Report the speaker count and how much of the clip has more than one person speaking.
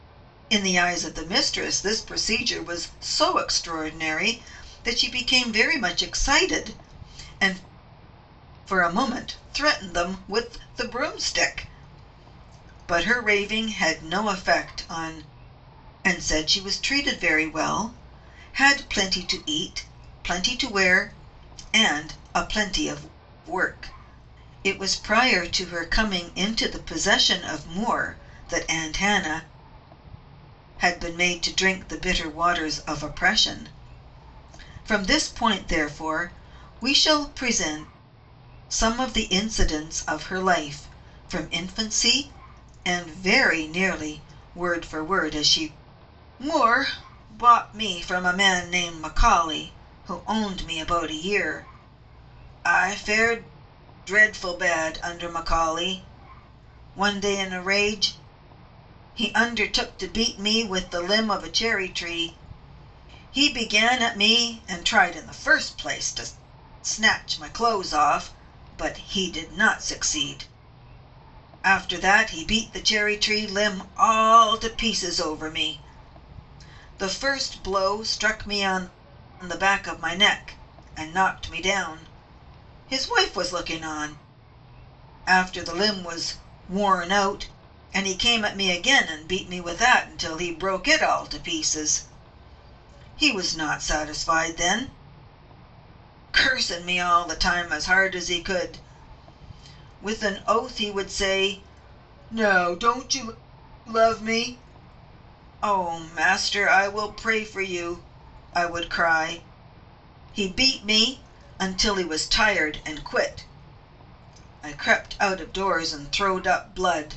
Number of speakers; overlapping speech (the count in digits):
1, no overlap